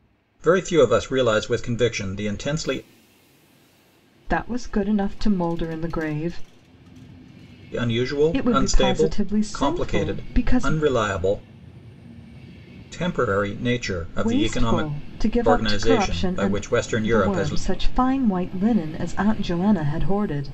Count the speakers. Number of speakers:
two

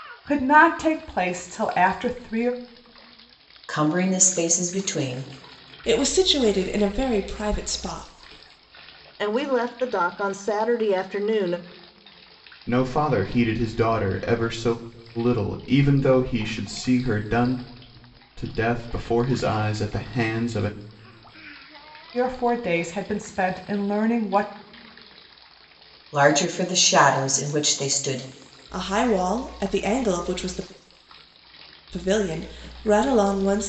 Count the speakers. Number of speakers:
five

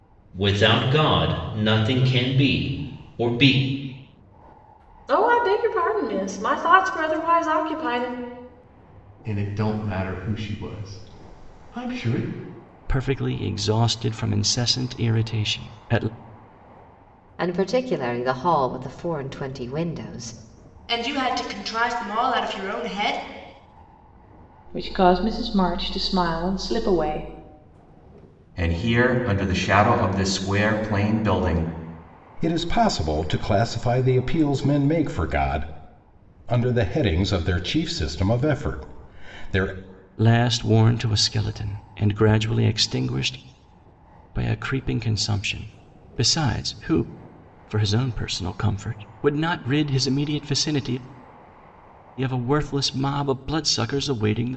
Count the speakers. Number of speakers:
nine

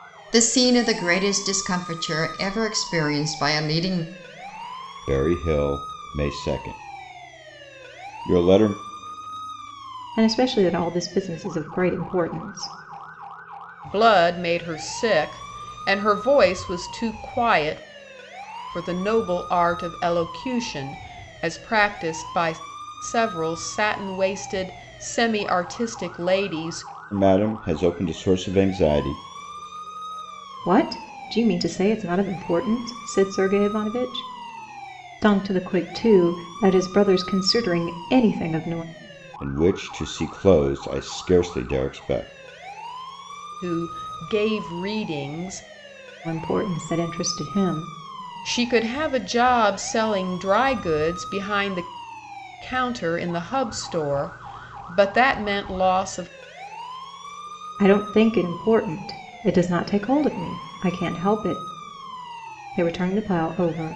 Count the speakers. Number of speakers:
four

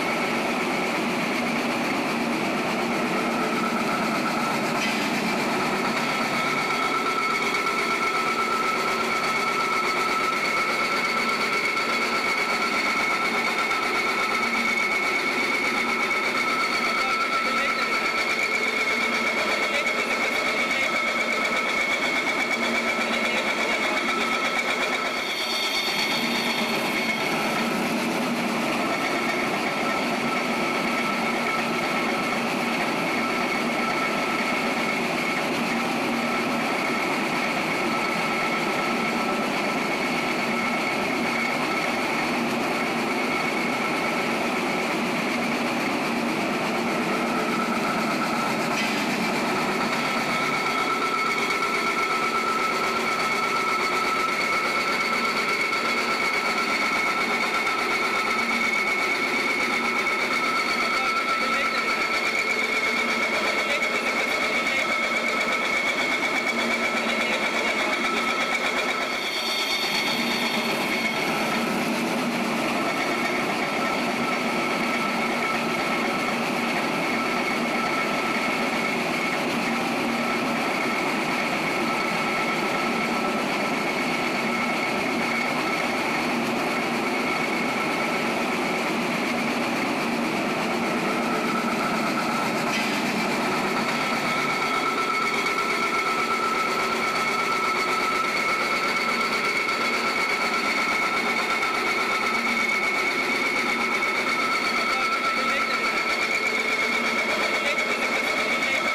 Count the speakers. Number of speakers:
zero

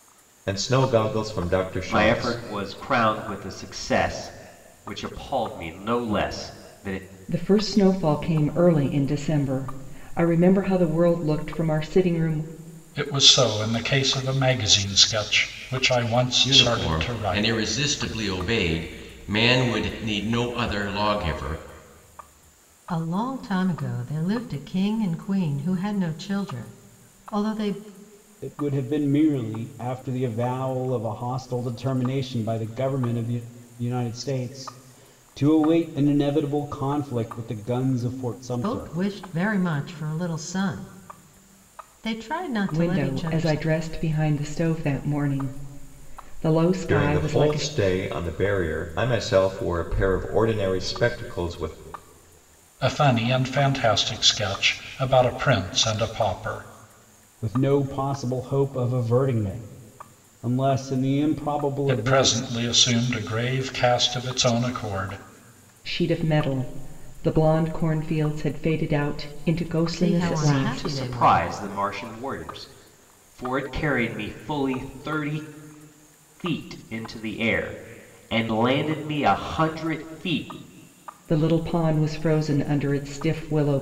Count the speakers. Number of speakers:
seven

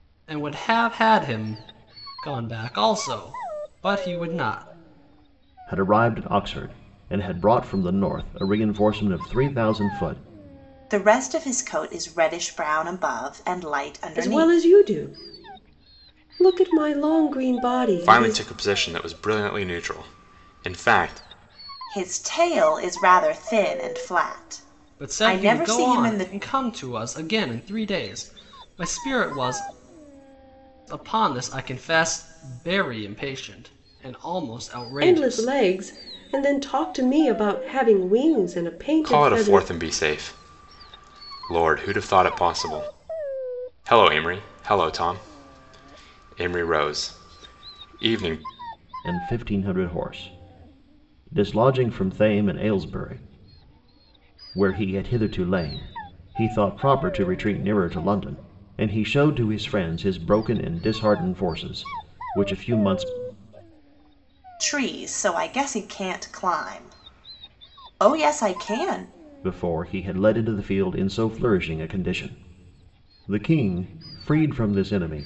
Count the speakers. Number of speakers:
five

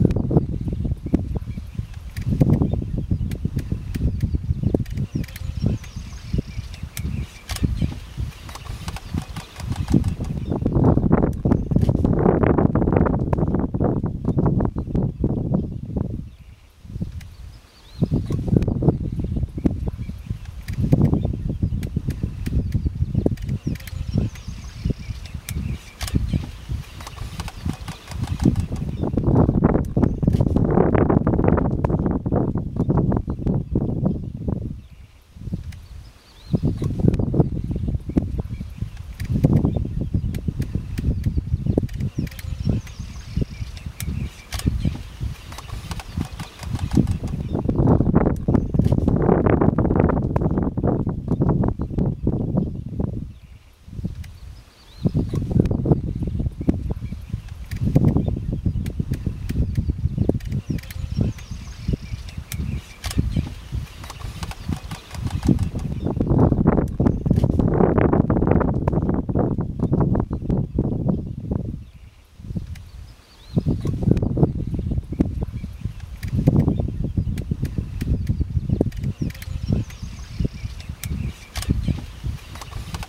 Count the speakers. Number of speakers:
zero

